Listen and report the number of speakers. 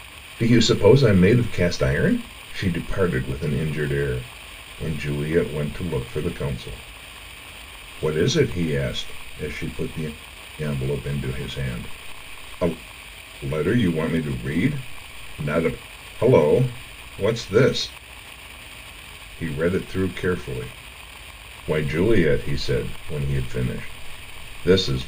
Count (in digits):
1